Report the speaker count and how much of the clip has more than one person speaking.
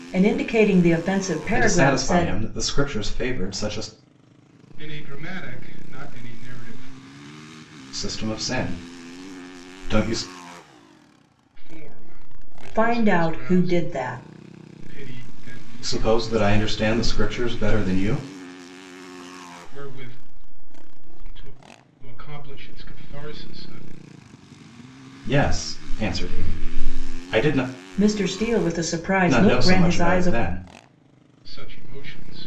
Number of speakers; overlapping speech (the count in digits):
3, about 11%